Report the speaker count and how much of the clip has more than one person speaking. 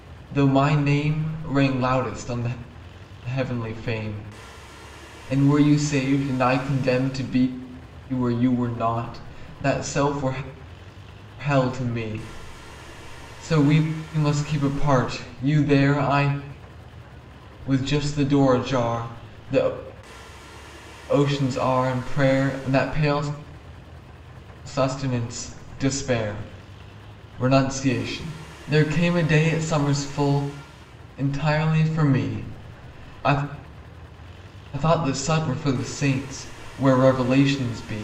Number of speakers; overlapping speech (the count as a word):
one, no overlap